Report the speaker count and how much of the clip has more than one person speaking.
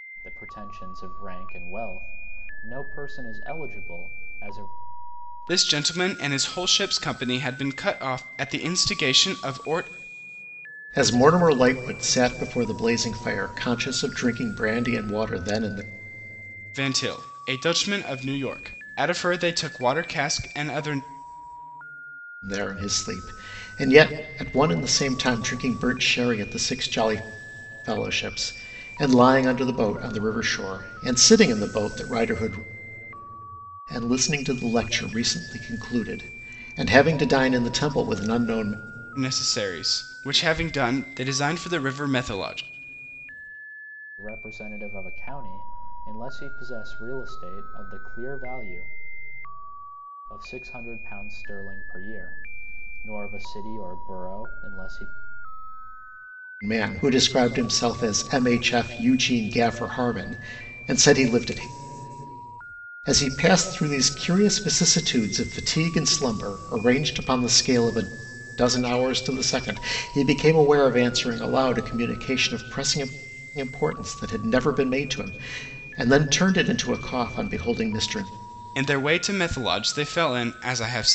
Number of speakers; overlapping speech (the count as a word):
three, no overlap